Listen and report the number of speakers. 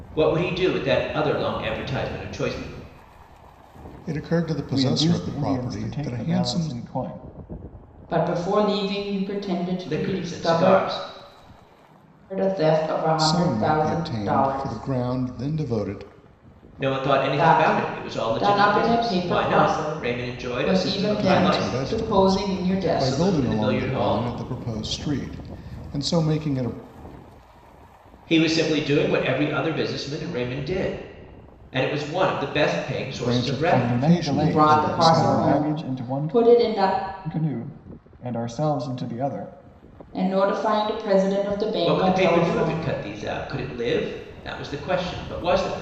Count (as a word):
four